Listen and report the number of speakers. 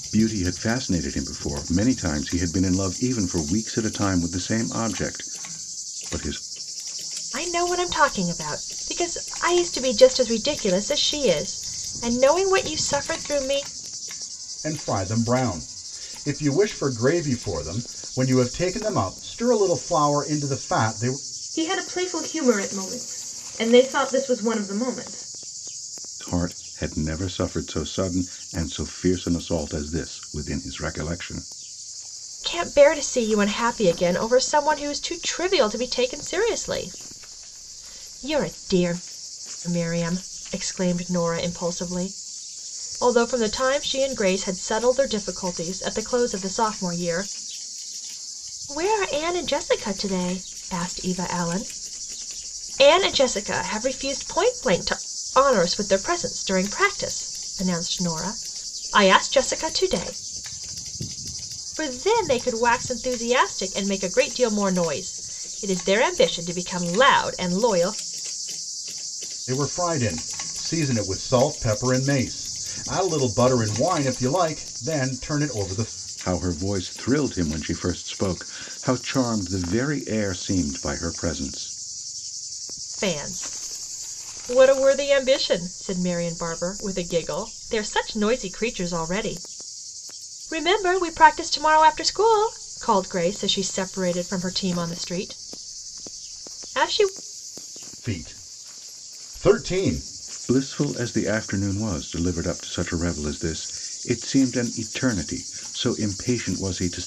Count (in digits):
4